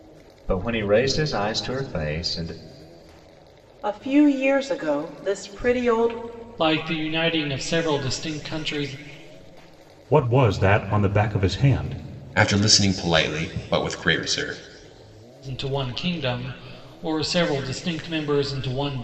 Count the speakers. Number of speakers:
5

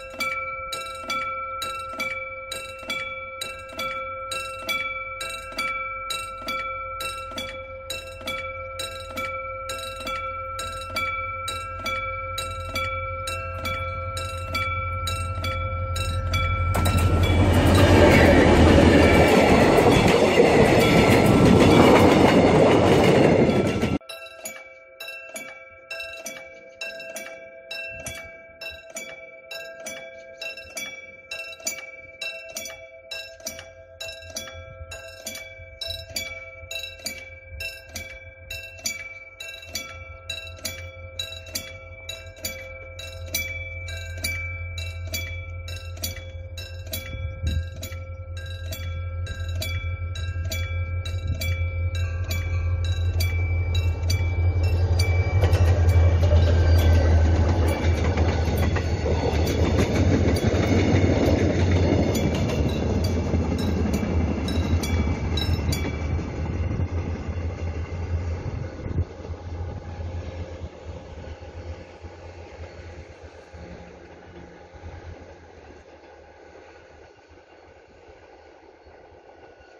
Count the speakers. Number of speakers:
0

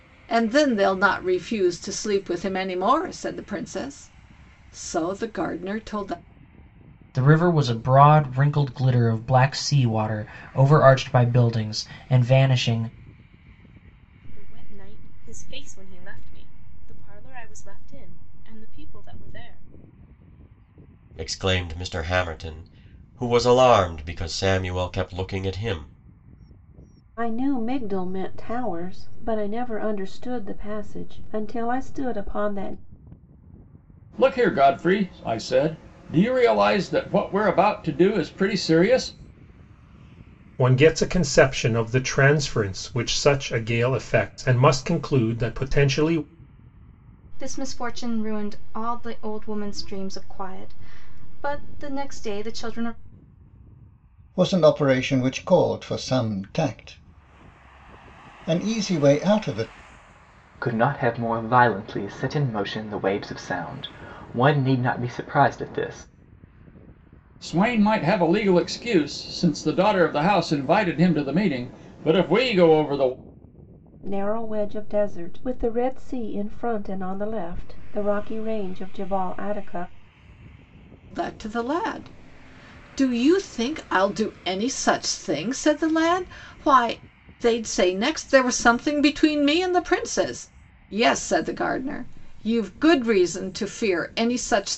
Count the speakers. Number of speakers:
10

